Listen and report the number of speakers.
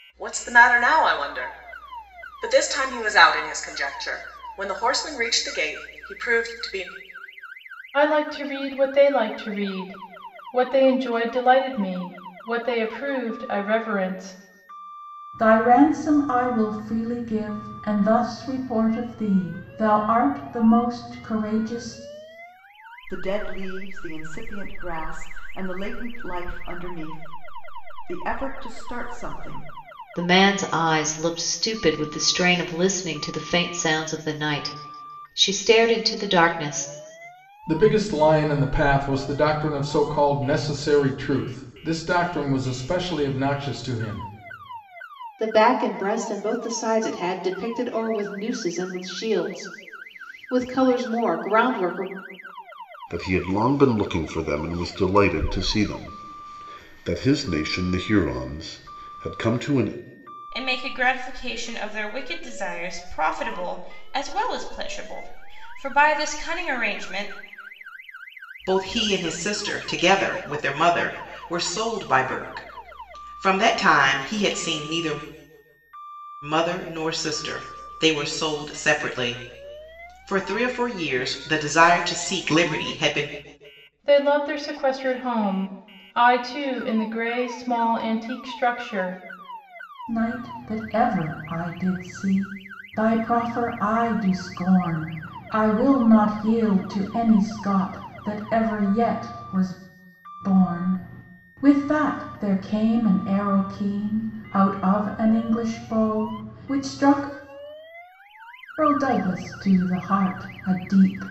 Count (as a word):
ten